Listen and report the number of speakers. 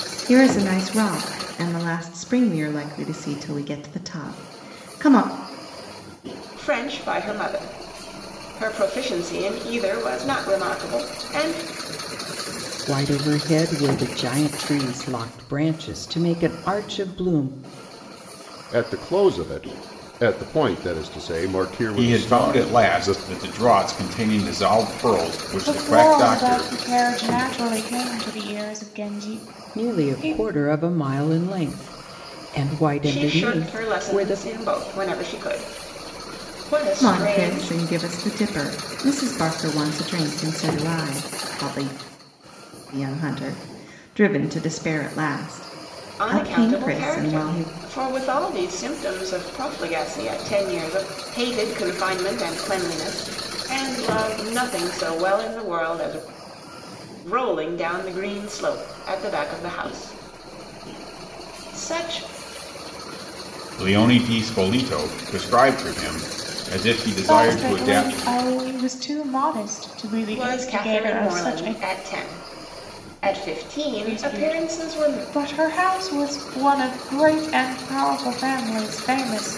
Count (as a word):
six